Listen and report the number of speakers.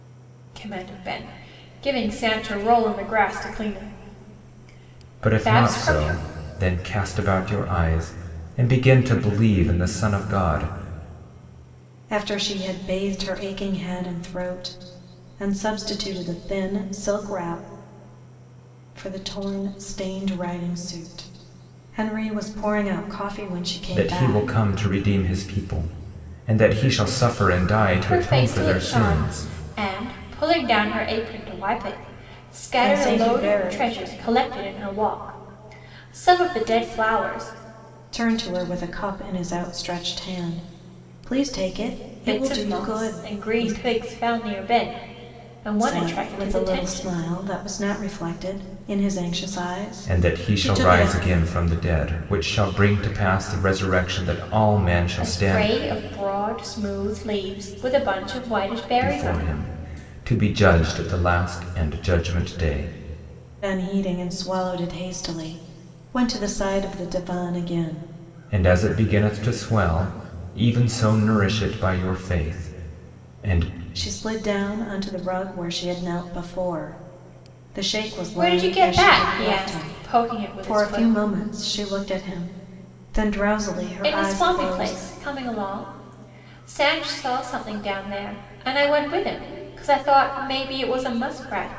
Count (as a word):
three